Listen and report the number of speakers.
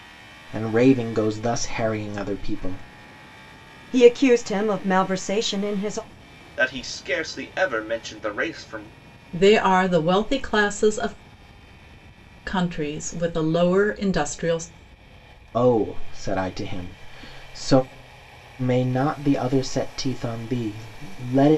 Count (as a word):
four